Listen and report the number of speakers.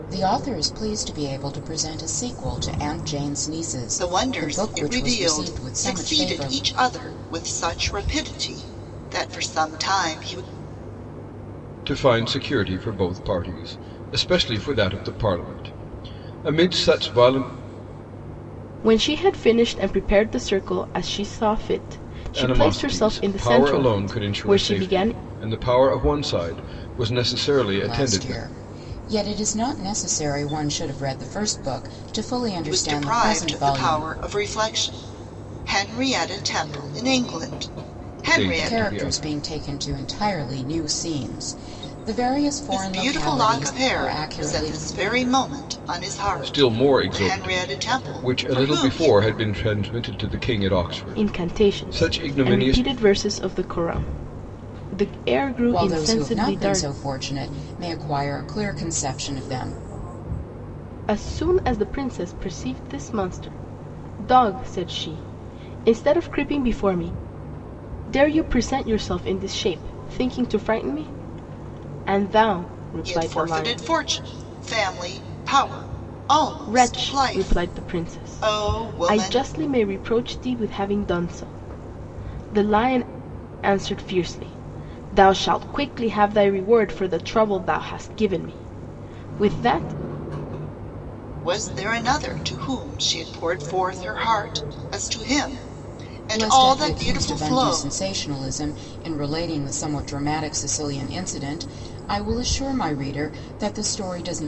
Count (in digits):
4